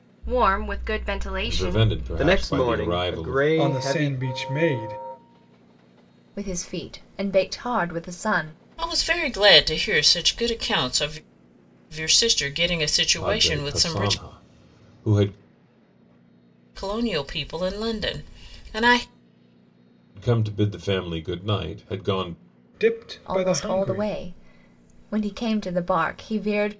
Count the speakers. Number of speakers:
6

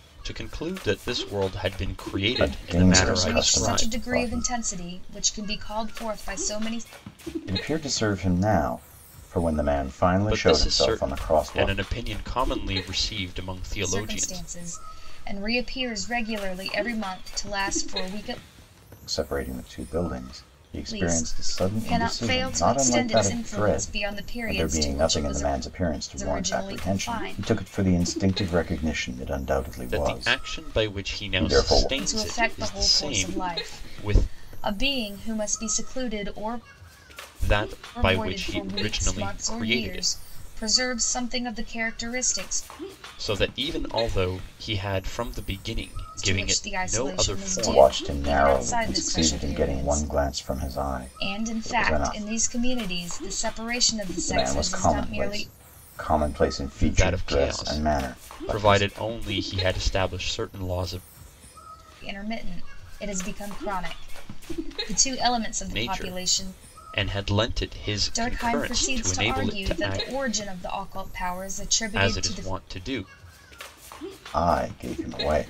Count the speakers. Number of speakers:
3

